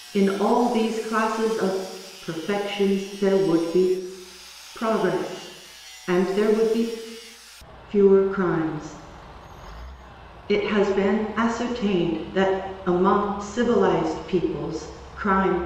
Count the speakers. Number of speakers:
one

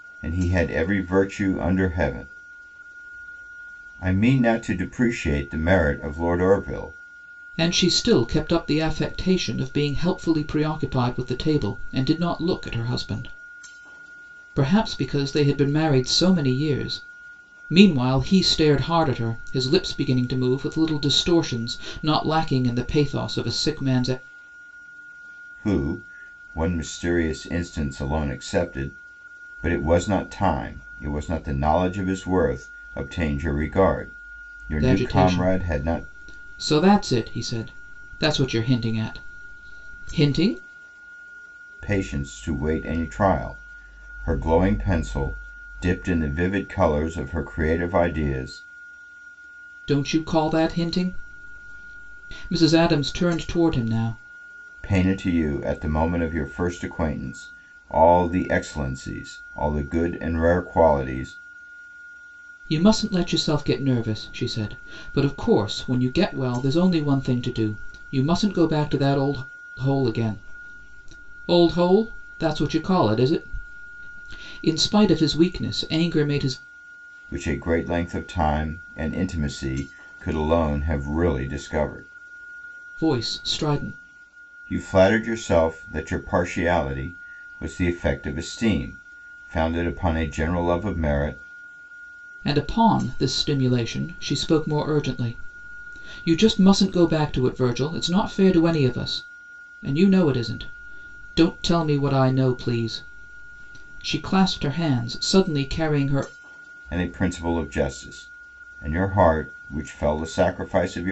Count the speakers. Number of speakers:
two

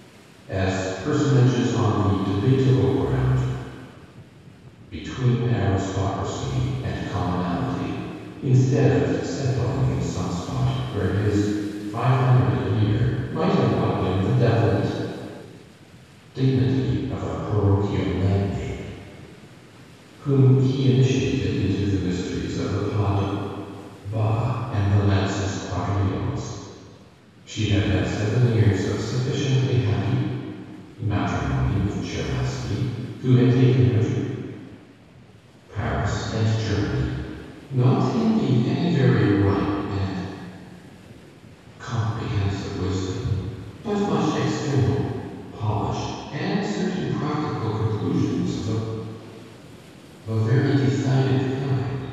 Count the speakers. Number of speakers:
one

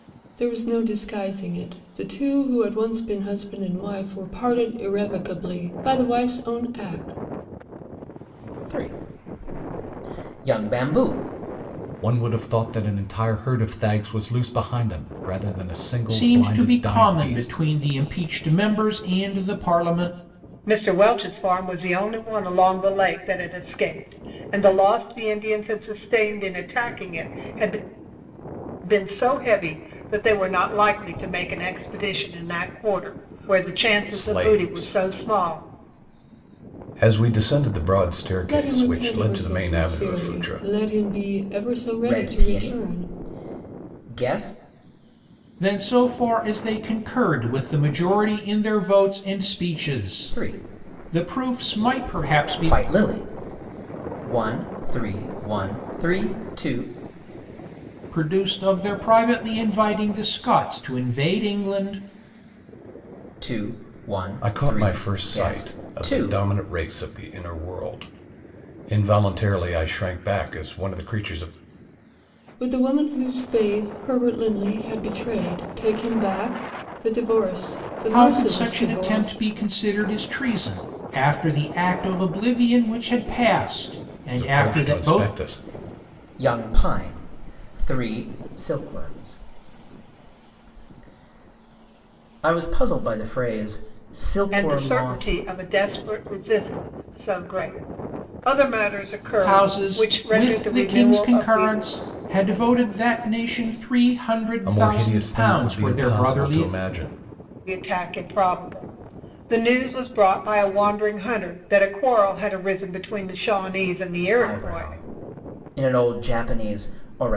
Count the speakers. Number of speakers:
five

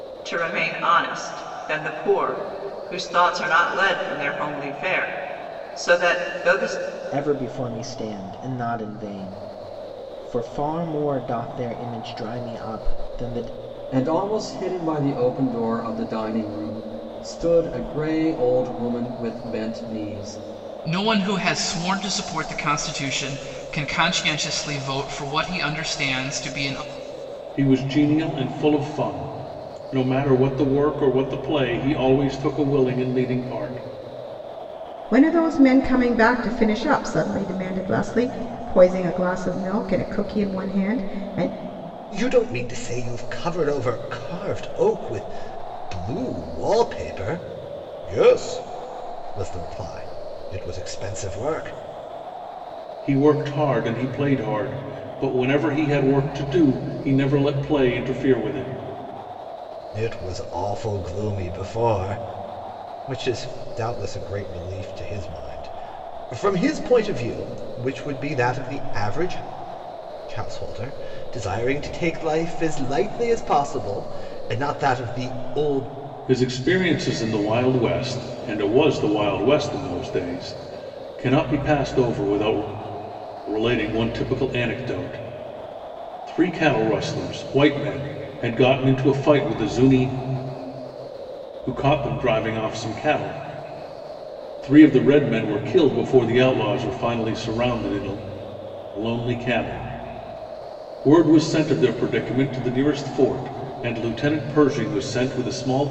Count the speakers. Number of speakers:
seven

